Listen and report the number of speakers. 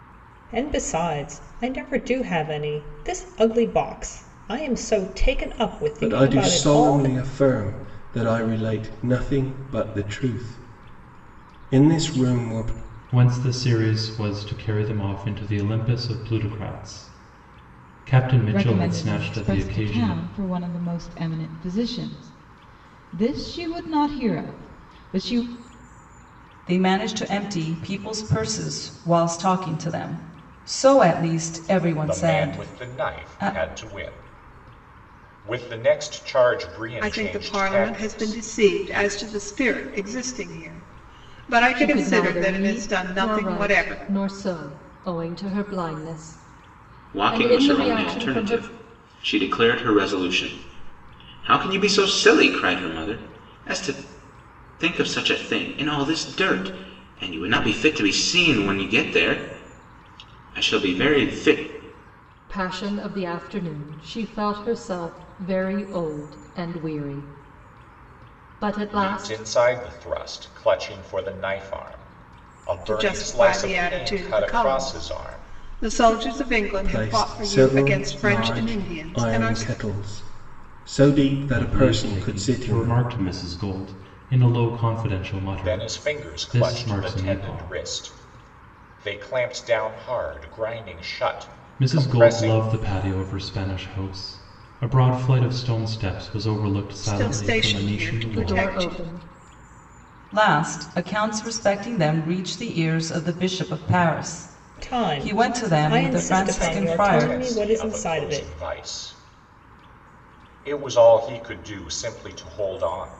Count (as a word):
nine